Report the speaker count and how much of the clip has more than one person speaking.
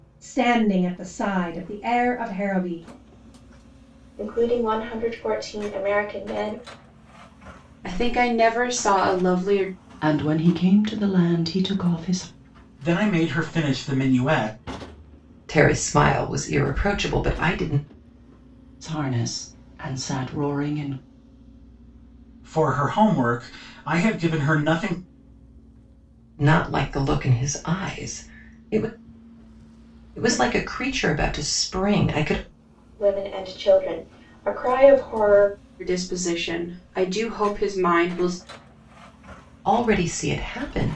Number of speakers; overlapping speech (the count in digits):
6, no overlap